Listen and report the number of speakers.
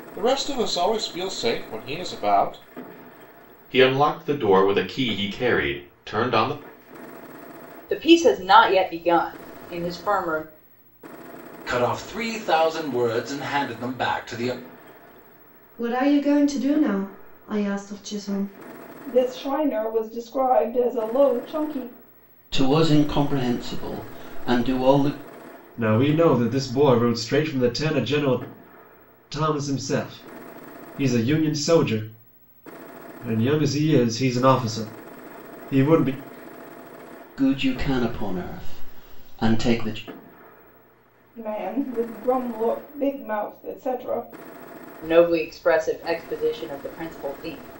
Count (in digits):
8